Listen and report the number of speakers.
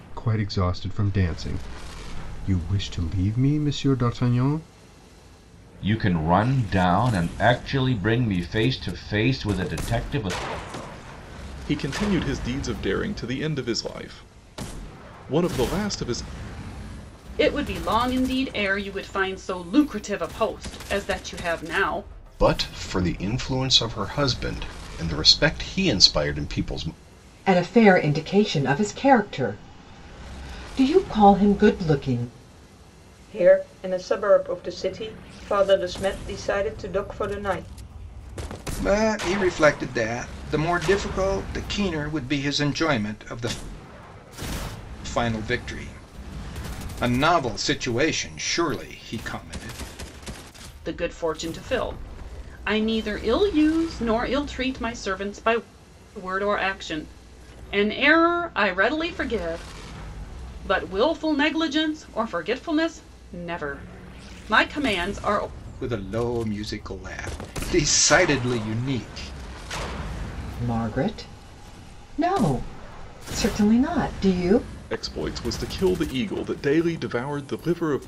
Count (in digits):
8